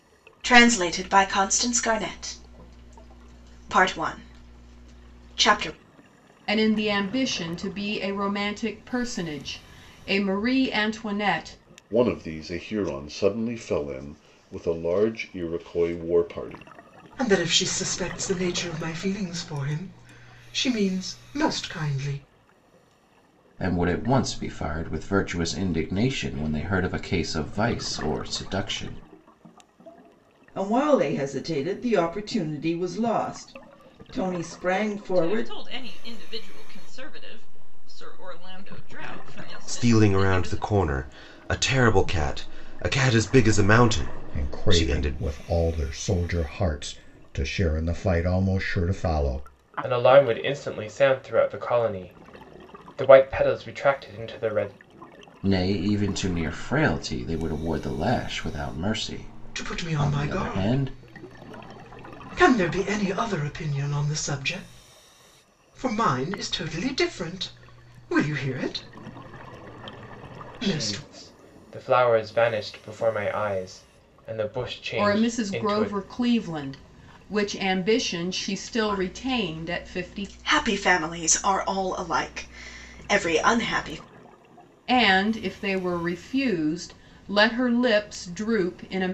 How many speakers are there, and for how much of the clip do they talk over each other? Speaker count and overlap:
10, about 8%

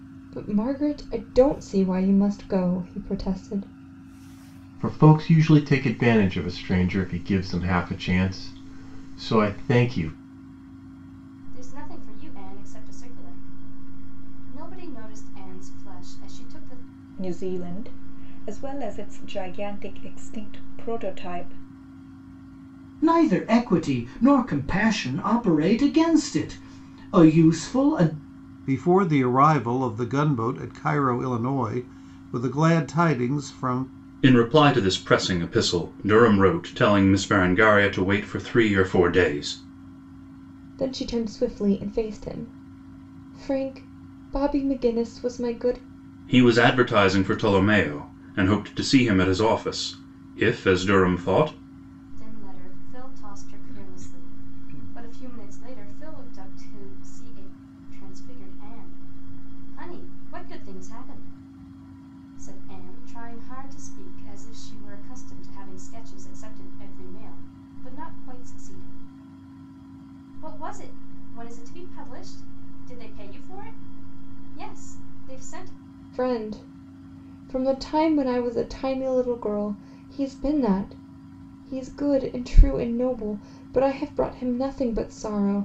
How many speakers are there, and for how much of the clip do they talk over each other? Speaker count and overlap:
7, no overlap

